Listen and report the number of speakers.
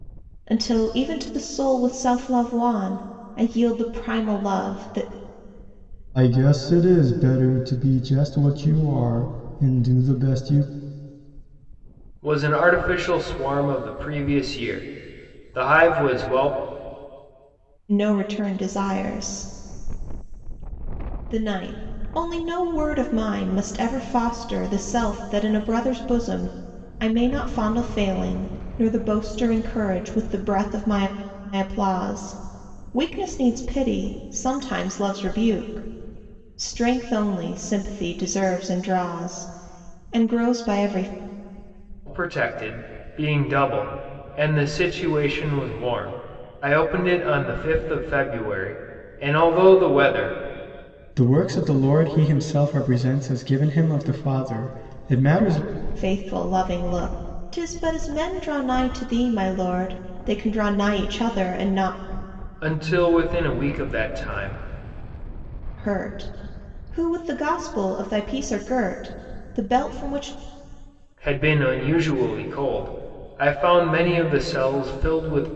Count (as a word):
three